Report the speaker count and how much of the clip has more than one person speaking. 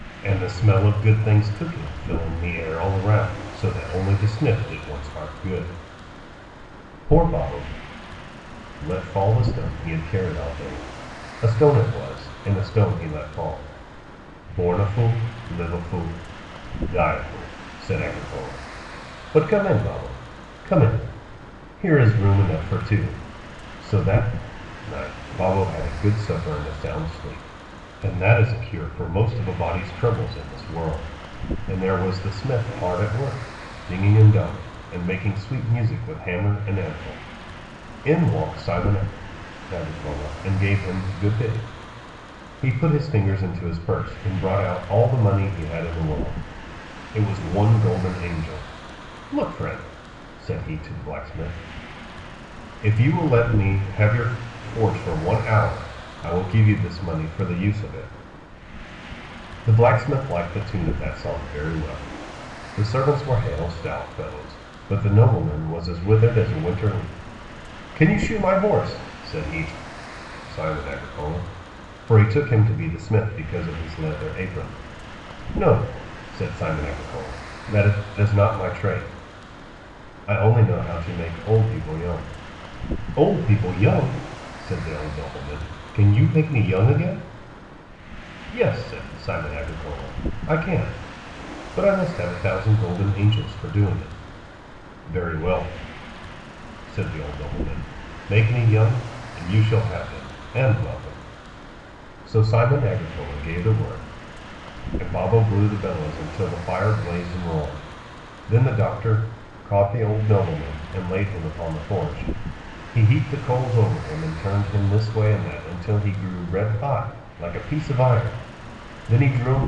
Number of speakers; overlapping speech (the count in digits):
1, no overlap